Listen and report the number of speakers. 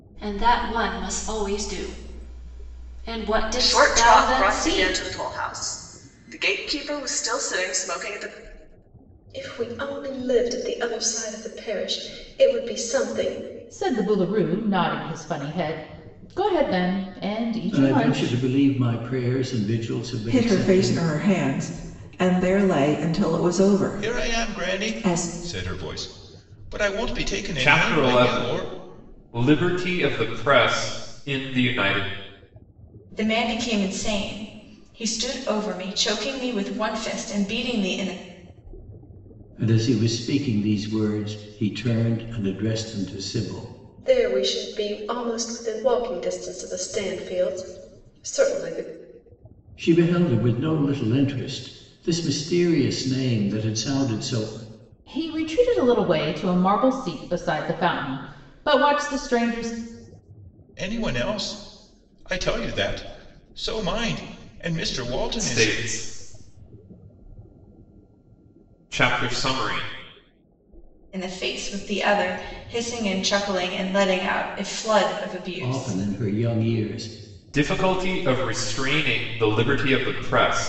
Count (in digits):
9